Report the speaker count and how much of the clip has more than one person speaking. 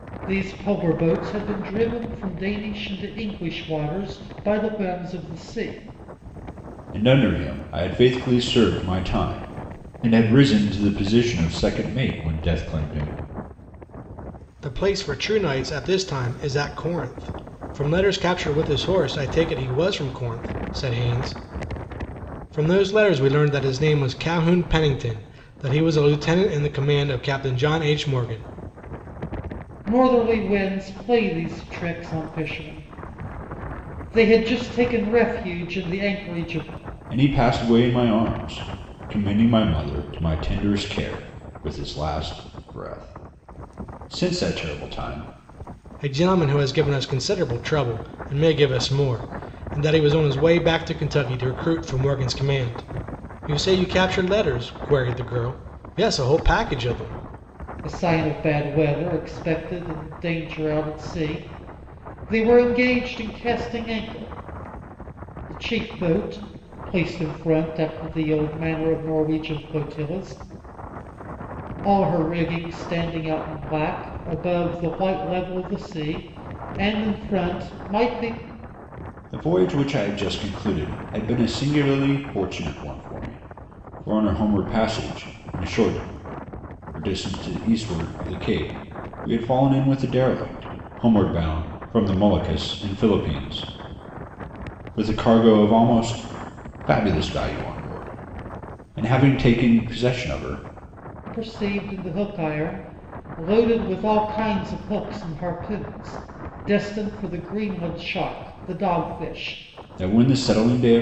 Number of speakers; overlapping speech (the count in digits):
3, no overlap